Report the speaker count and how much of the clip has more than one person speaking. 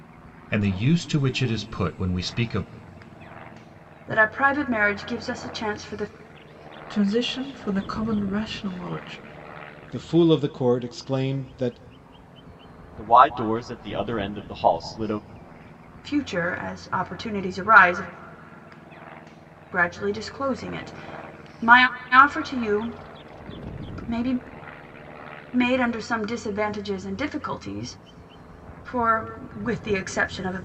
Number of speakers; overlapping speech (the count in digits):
5, no overlap